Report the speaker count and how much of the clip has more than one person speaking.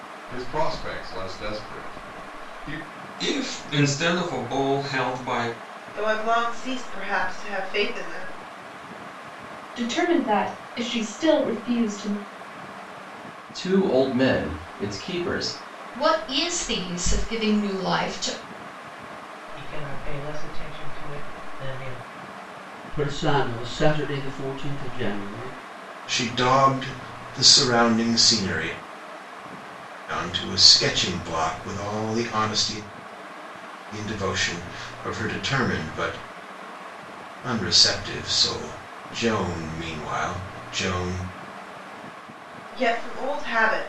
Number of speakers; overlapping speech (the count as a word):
nine, no overlap